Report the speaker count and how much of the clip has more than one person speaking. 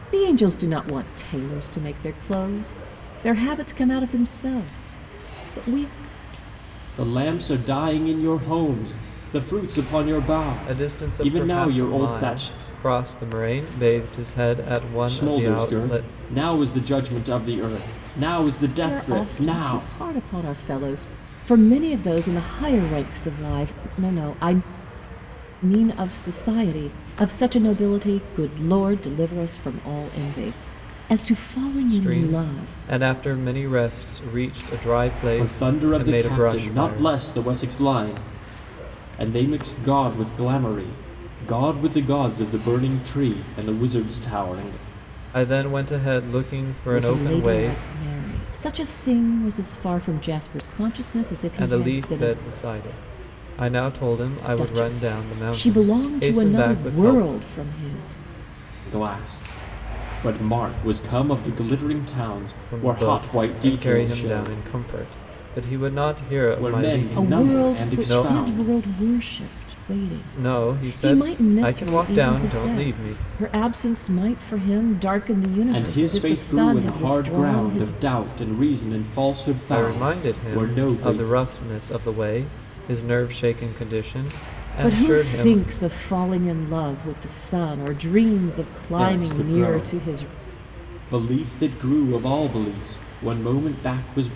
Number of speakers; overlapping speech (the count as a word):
three, about 26%